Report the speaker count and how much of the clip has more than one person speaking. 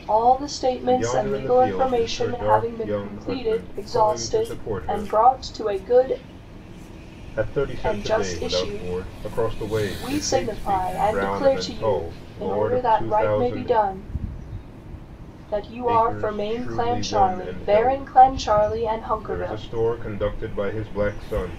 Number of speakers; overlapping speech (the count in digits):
2, about 59%